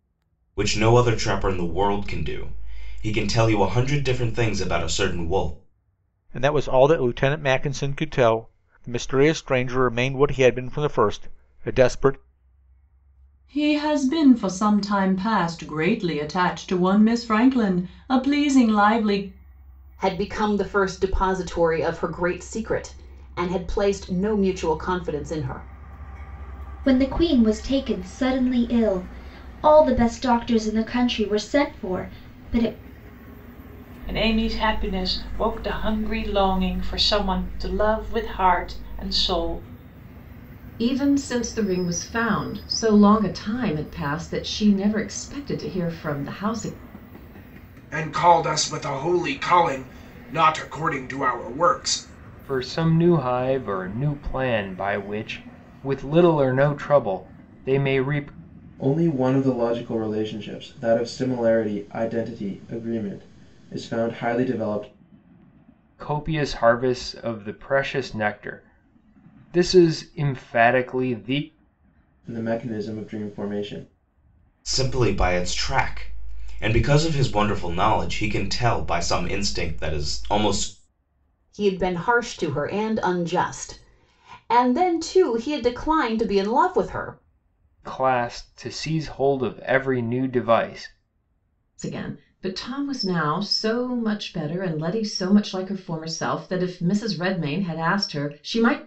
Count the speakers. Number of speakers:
ten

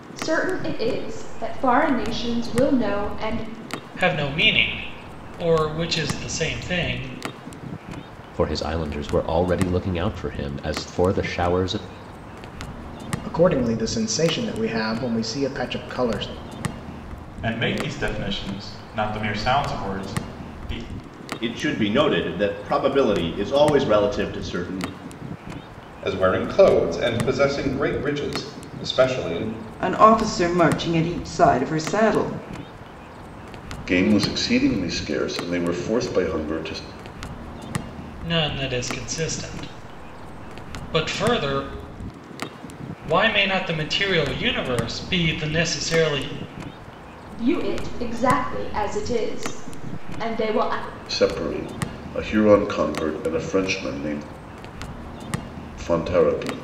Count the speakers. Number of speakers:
nine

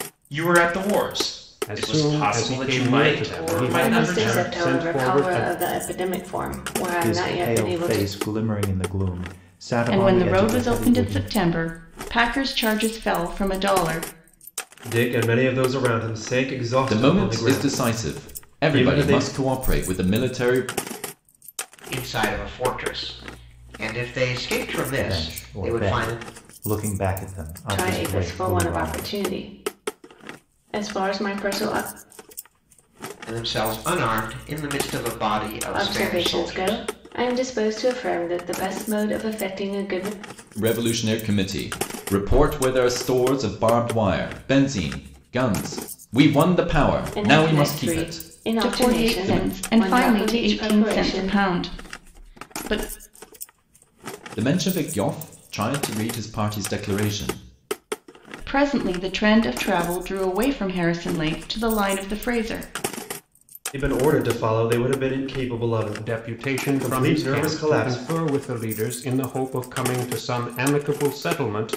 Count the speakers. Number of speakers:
eight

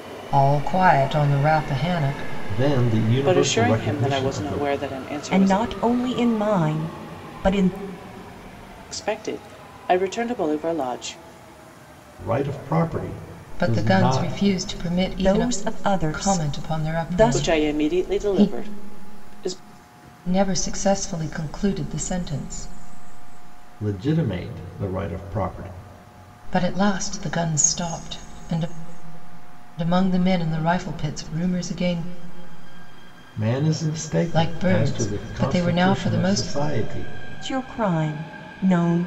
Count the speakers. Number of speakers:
four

